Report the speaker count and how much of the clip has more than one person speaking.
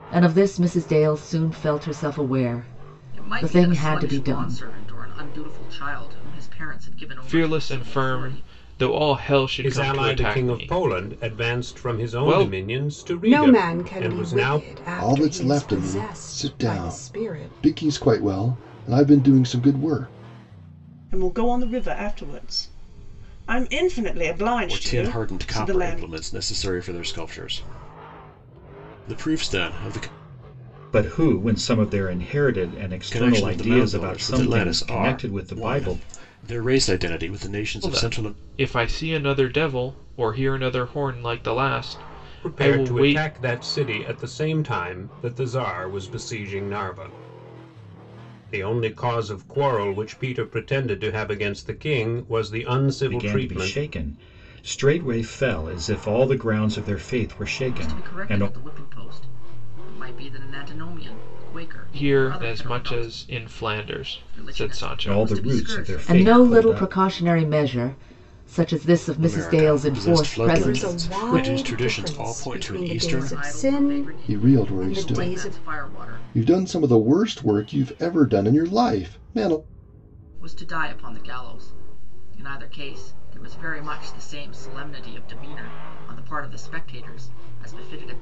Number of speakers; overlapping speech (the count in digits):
9, about 32%